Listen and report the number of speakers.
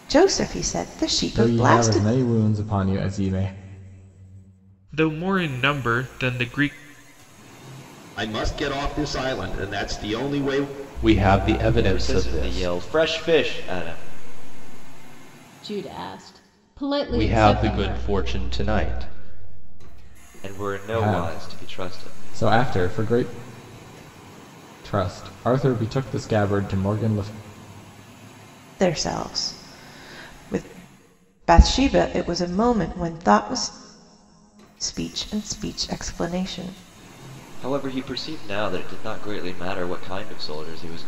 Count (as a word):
seven